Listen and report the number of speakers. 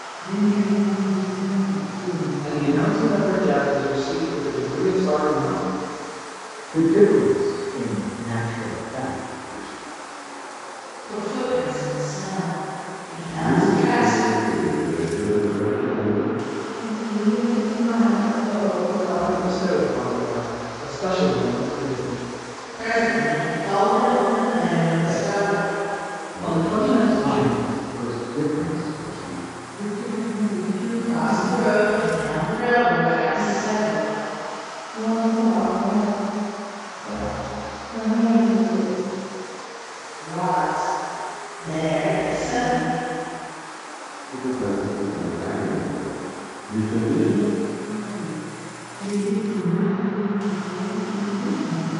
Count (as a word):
six